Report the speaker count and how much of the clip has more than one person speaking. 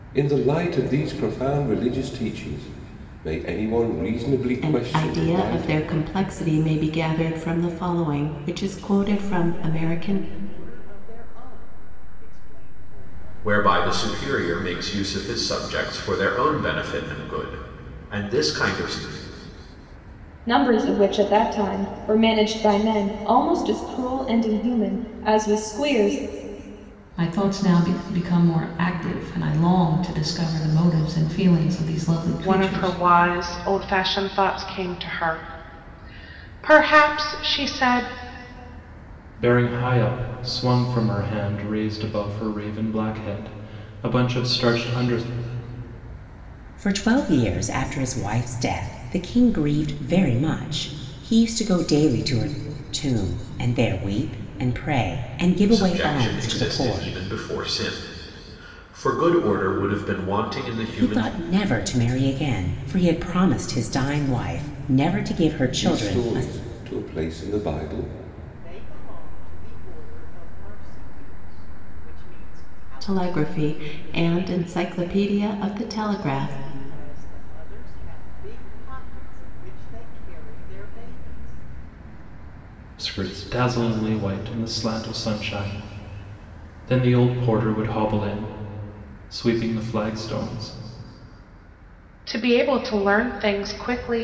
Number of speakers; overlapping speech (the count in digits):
9, about 9%